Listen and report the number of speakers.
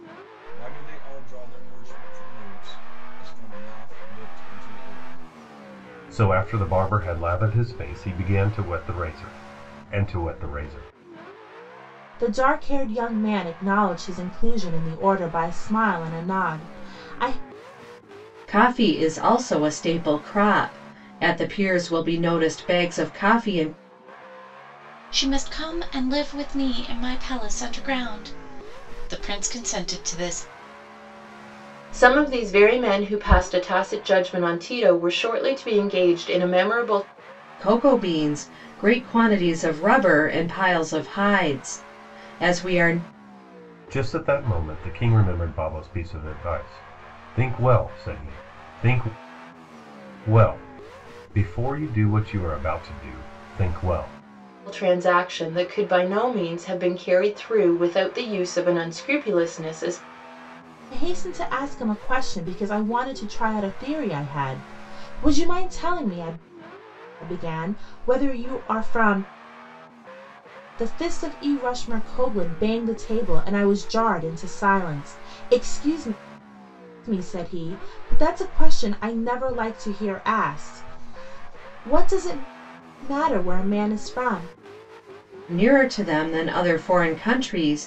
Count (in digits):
6